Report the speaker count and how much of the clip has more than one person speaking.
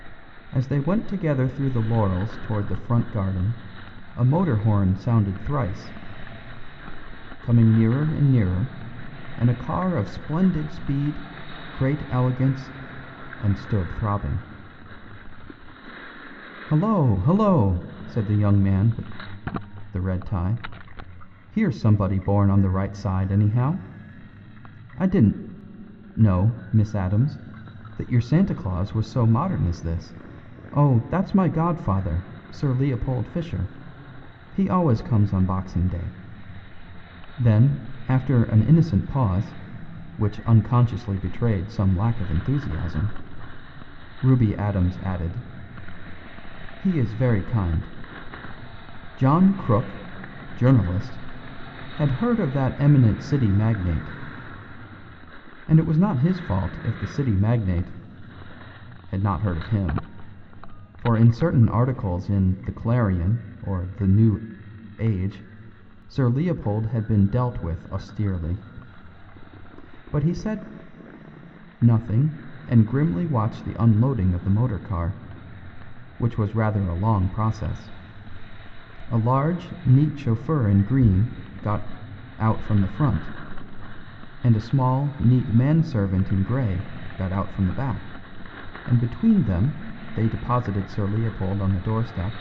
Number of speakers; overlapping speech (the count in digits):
1, no overlap